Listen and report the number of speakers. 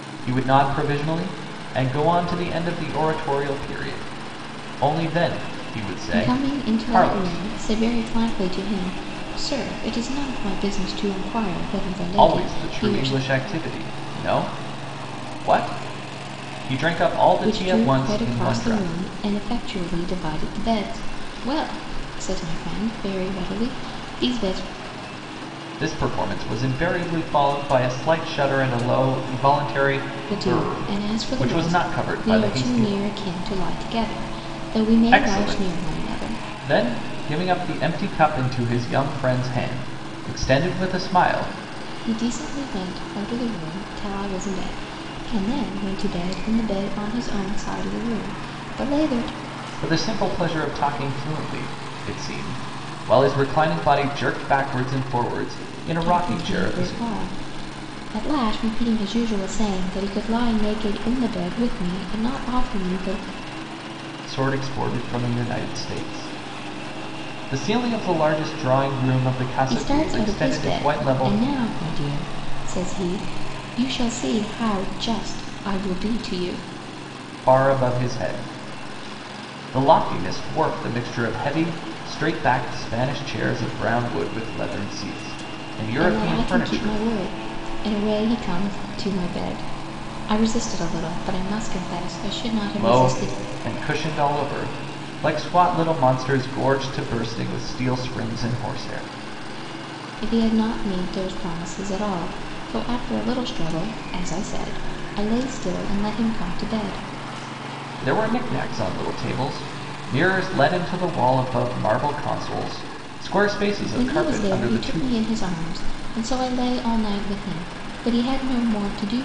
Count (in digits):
2